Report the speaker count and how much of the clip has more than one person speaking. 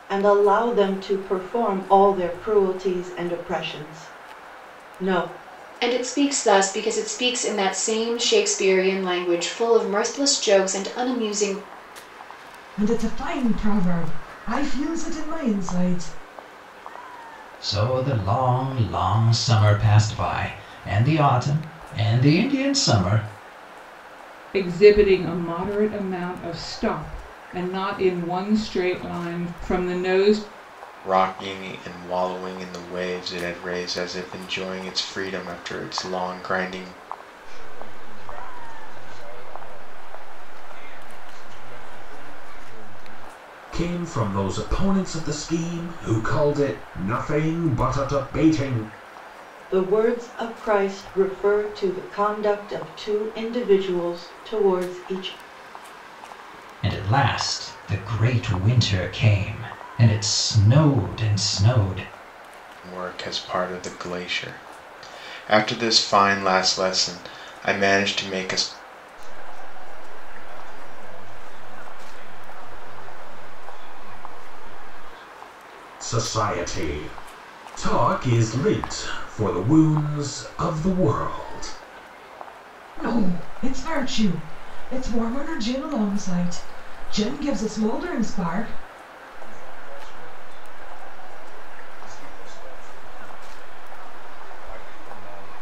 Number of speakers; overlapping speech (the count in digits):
8, no overlap